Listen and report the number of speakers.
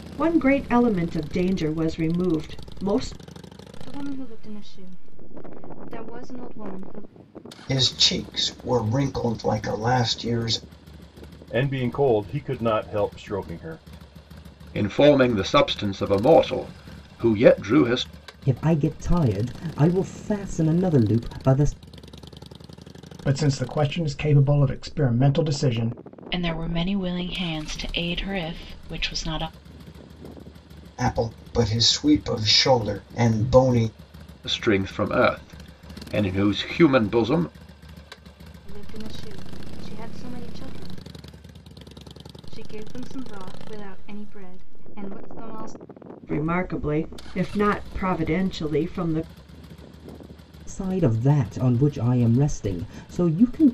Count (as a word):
eight